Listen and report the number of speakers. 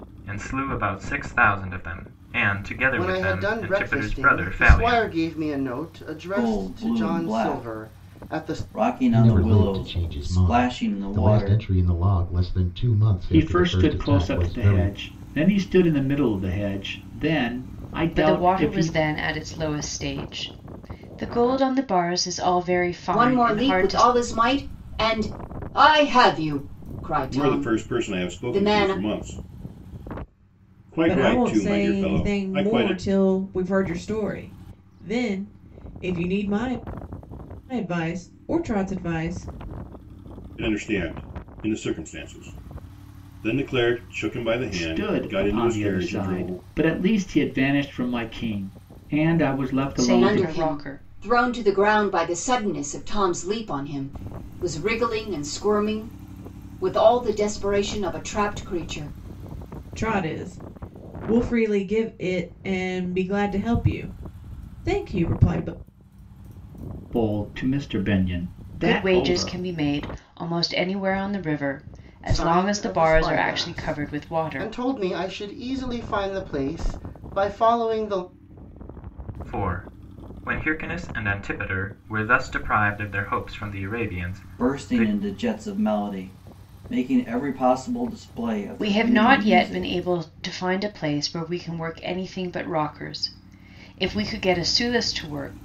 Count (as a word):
nine